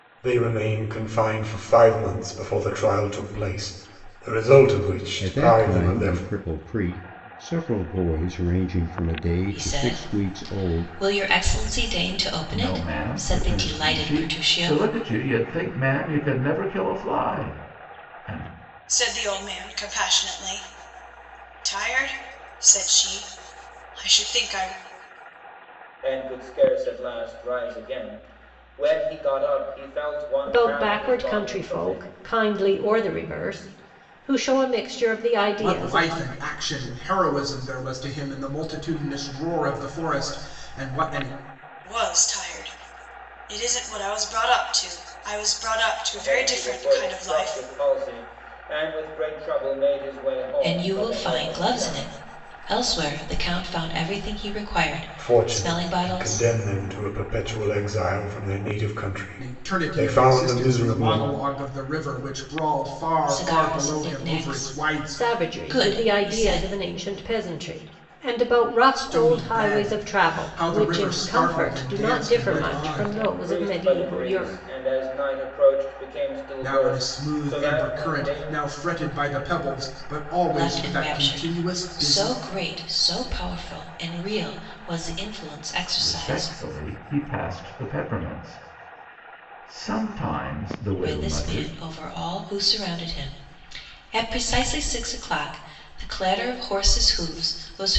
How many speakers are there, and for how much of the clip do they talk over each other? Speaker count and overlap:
8, about 28%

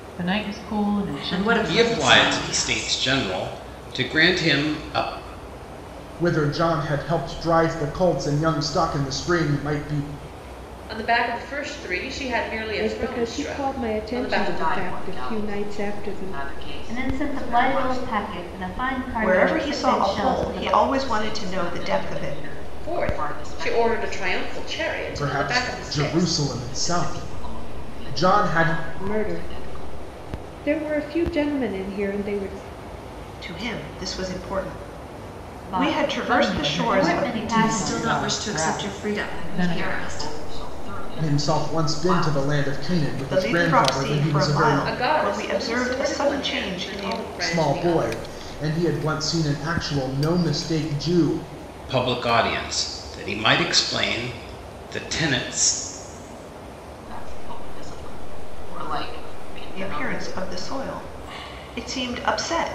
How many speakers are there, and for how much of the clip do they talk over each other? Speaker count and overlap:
9, about 46%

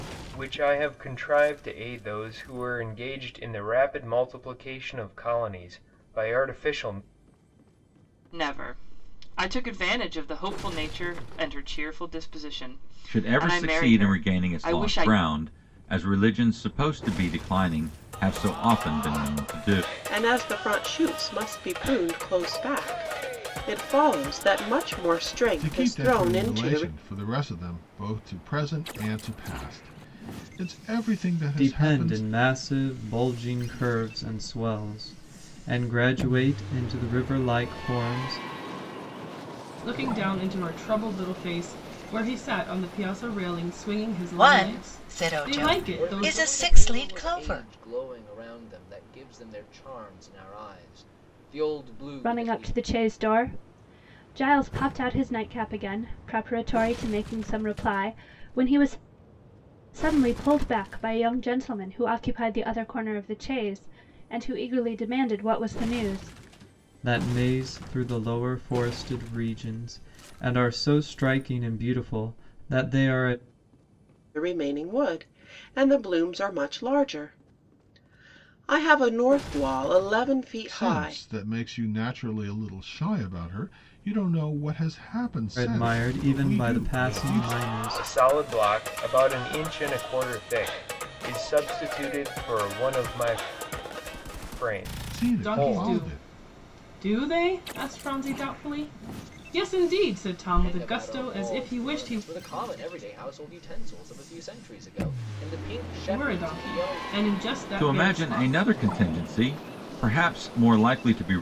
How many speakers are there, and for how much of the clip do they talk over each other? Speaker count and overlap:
10, about 14%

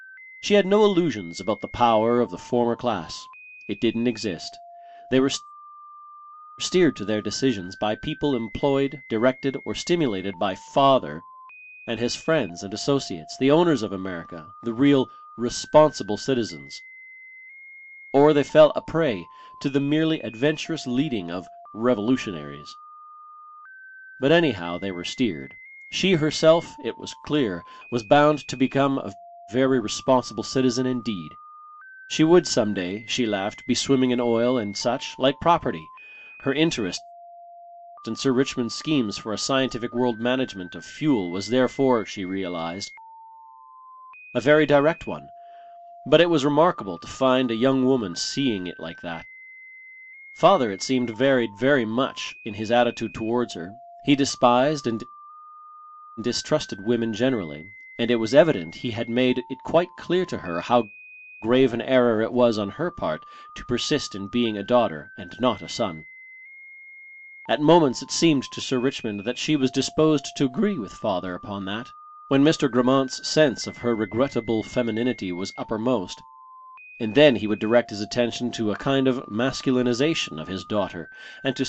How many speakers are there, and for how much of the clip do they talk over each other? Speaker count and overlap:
1, no overlap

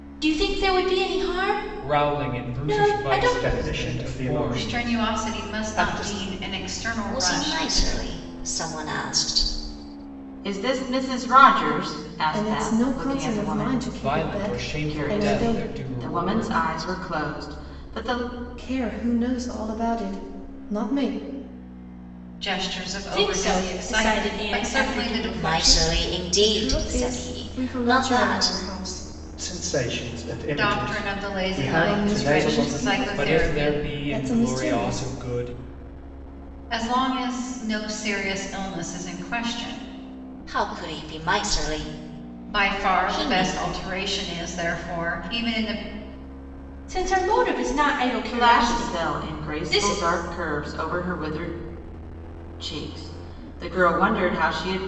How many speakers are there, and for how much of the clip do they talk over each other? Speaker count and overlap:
7, about 40%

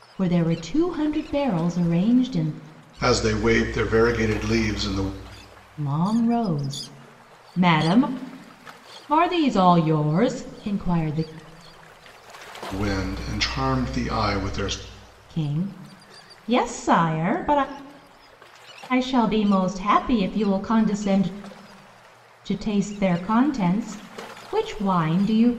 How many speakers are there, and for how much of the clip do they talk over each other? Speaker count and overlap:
2, no overlap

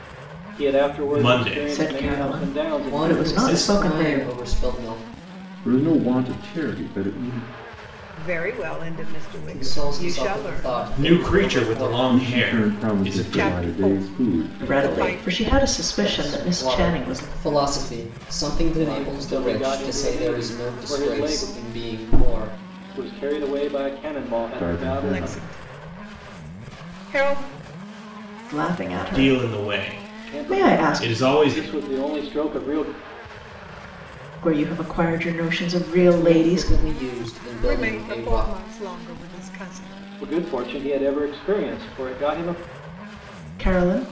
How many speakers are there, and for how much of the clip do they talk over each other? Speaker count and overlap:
6, about 42%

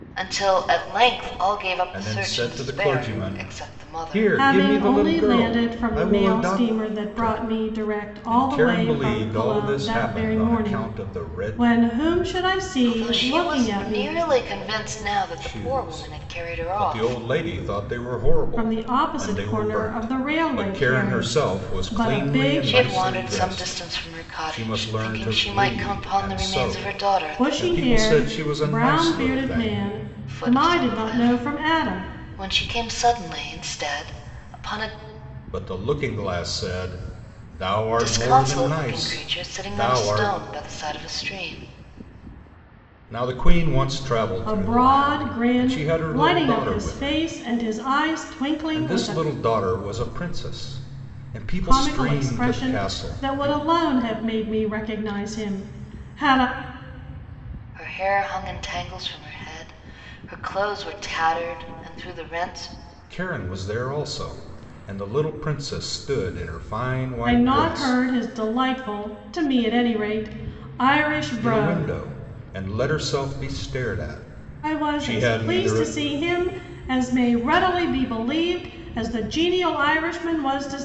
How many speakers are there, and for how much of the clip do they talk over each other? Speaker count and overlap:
3, about 44%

